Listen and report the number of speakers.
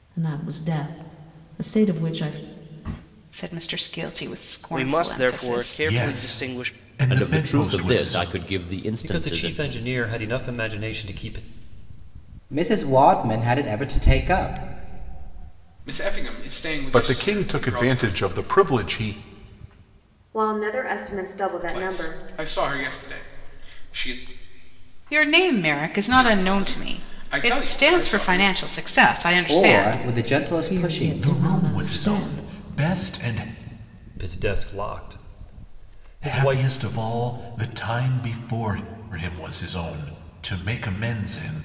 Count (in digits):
10